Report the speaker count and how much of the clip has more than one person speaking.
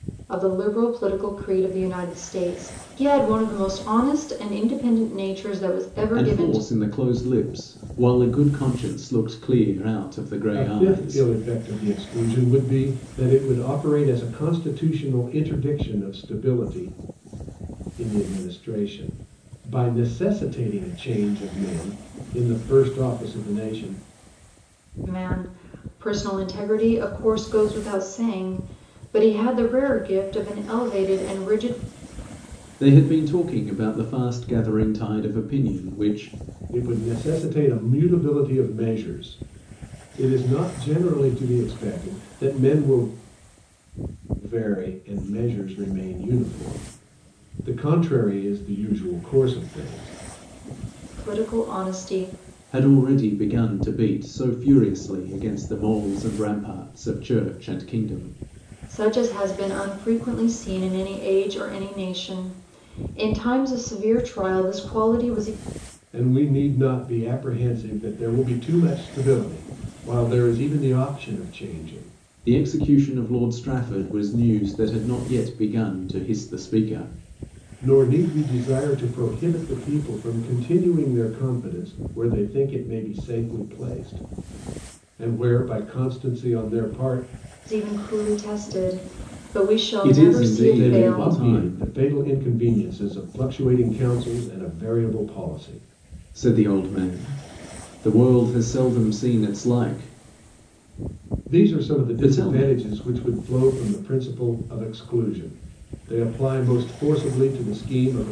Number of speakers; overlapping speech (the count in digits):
3, about 4%